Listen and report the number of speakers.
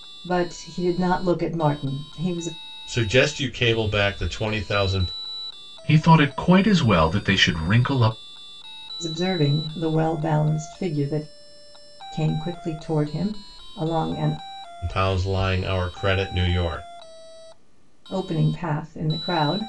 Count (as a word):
three